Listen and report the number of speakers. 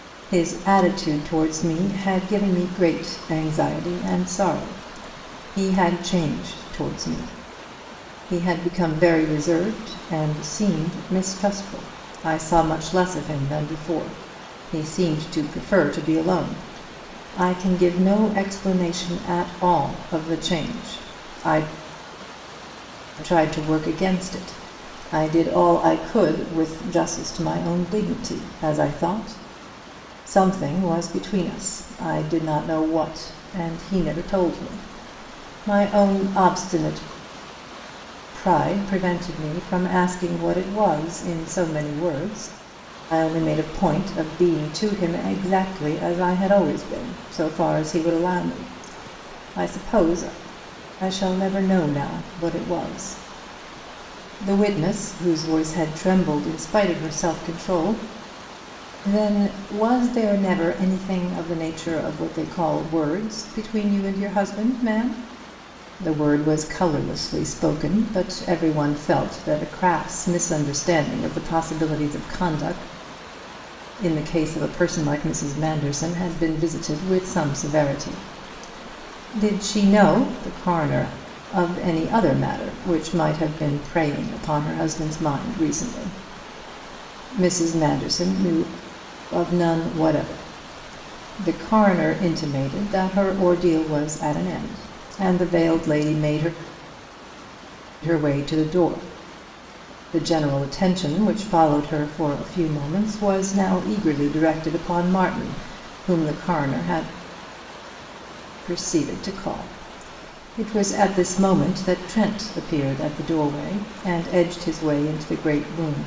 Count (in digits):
1